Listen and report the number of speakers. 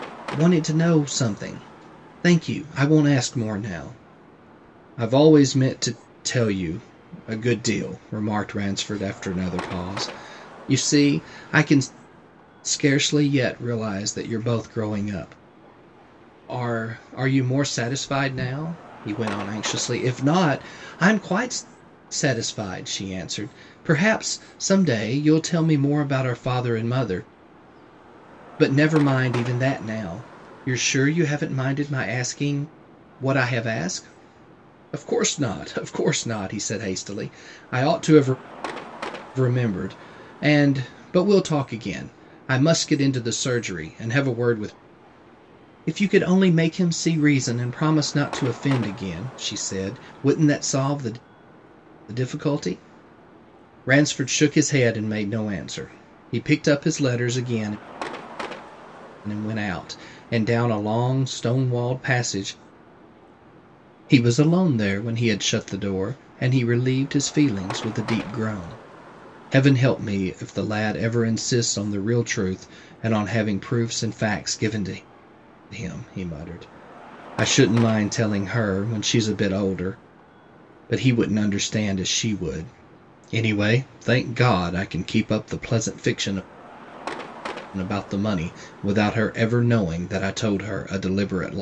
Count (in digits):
1